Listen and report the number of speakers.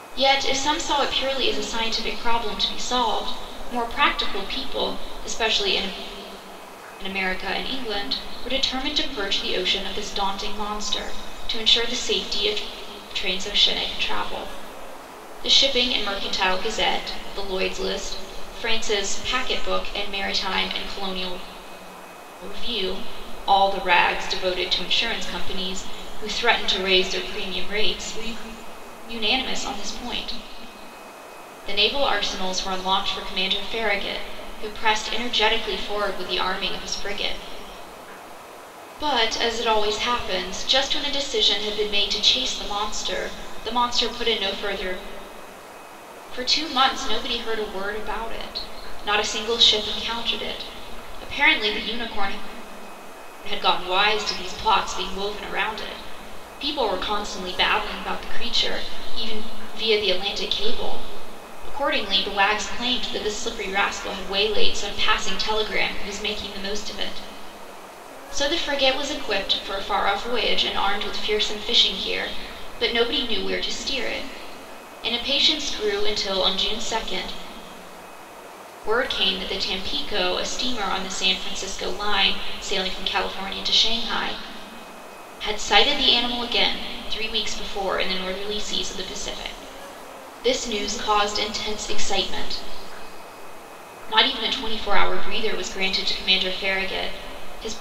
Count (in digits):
1